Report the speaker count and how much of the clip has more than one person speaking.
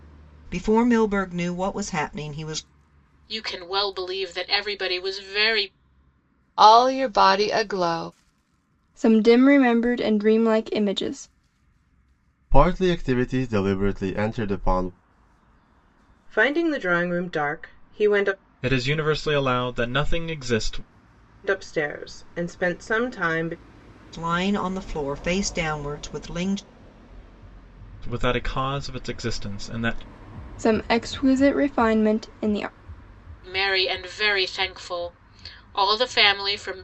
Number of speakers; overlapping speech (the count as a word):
seven, no overlap